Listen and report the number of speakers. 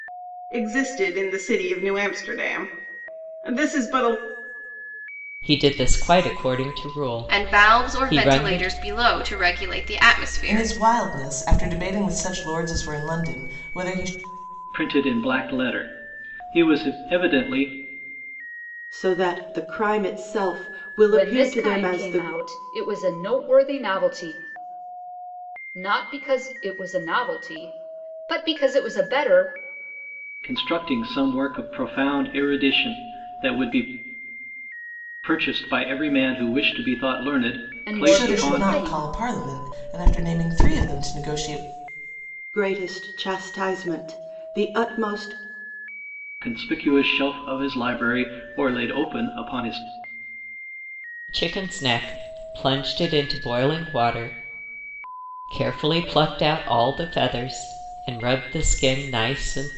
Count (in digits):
7